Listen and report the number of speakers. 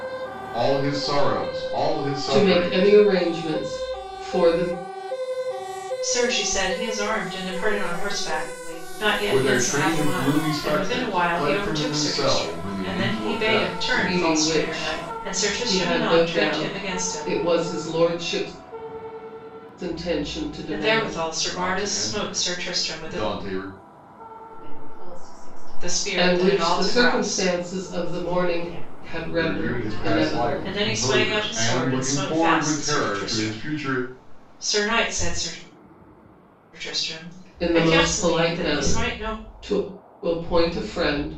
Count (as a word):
four